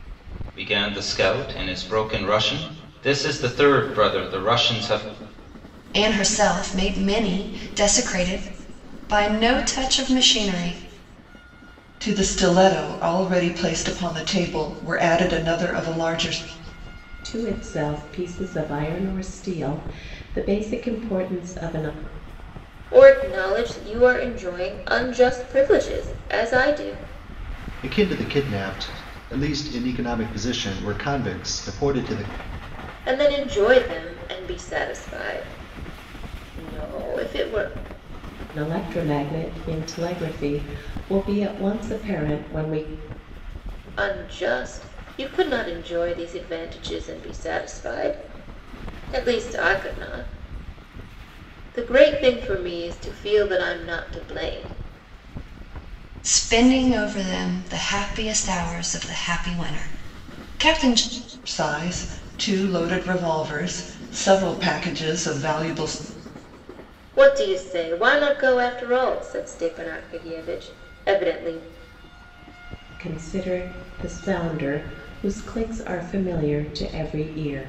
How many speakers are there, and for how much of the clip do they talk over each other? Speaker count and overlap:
6, no overlap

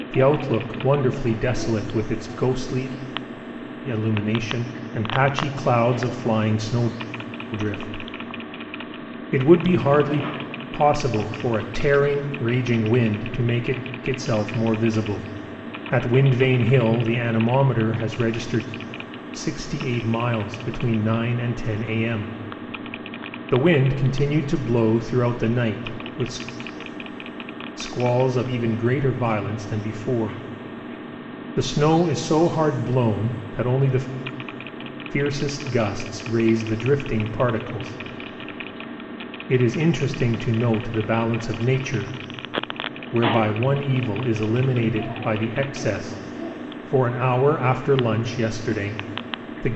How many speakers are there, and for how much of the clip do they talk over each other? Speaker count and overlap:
1, no overlap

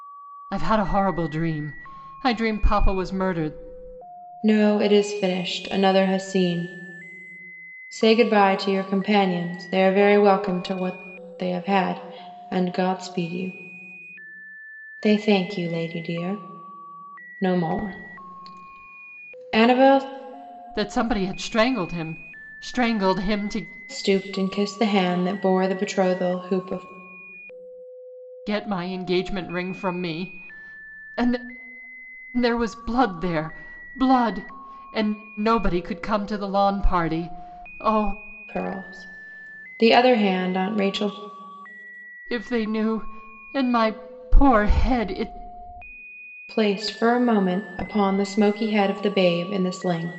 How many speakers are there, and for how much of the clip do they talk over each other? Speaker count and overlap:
2, no overlap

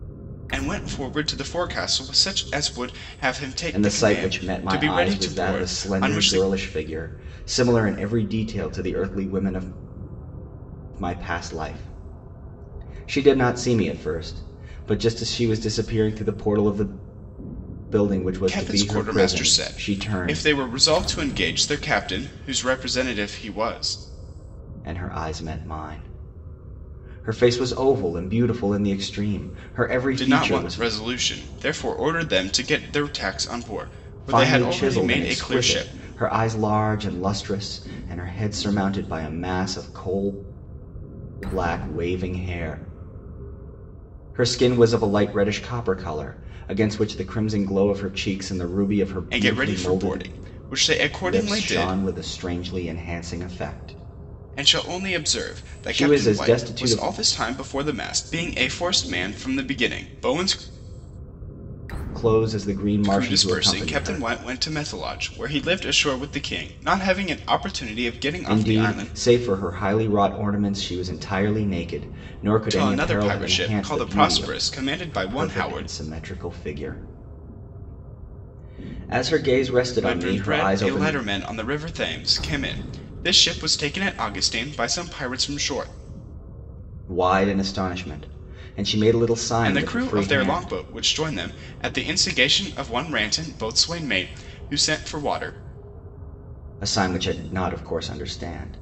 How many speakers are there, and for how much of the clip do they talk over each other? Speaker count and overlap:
2, about 19%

